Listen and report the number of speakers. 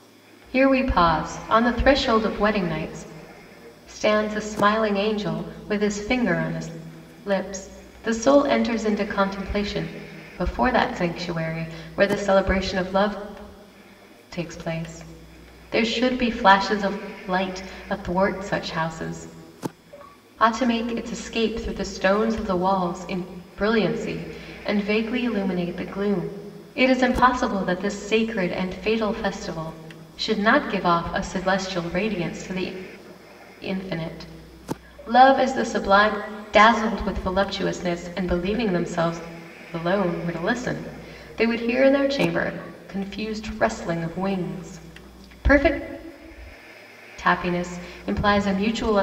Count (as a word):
one